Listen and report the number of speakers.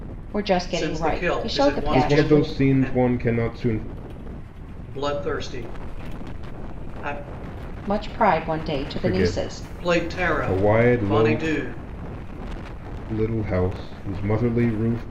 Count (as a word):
three